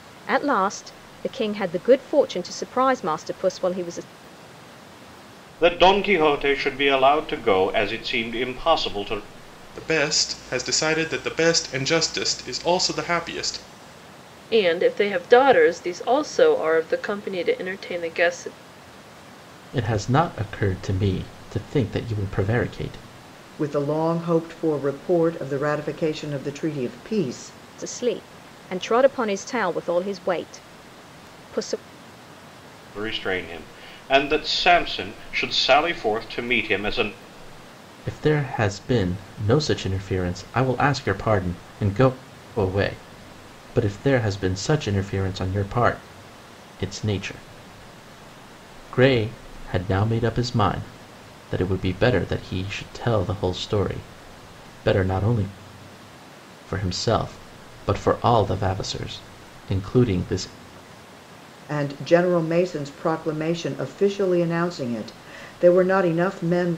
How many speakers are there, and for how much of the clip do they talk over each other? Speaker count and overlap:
6, no overlap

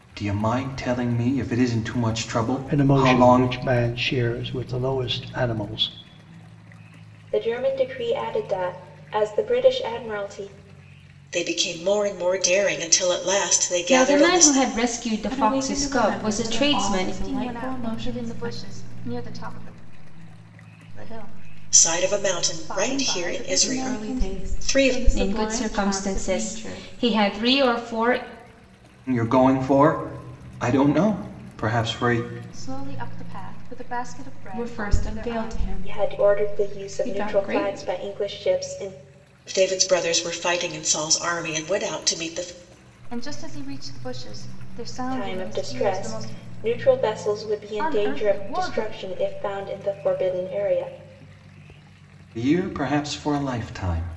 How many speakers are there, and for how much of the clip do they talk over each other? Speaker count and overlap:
7, about 29%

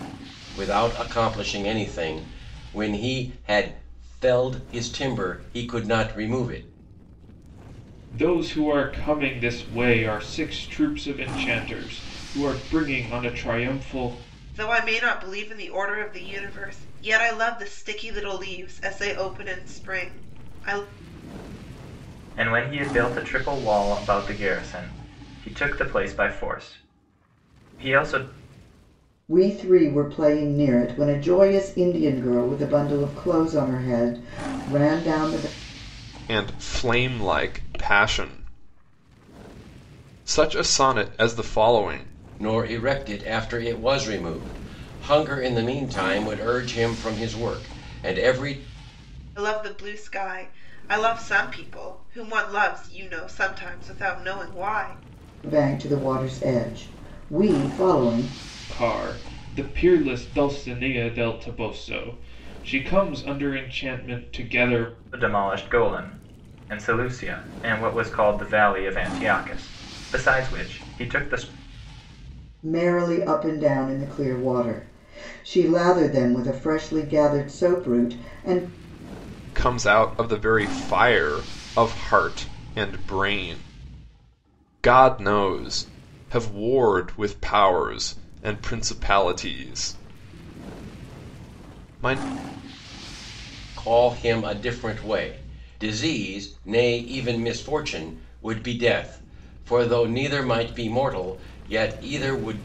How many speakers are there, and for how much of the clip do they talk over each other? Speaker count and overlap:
6, no overlap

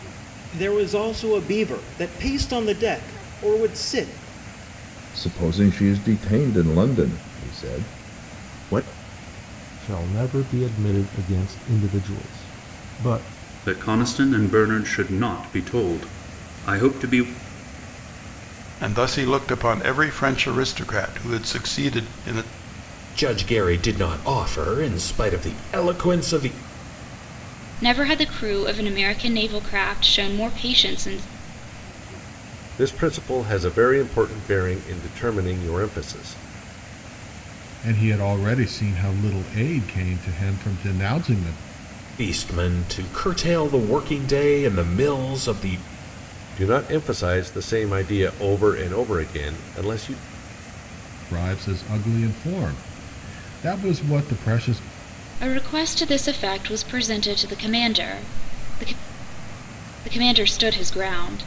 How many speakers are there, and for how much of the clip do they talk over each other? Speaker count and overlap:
9, no overlap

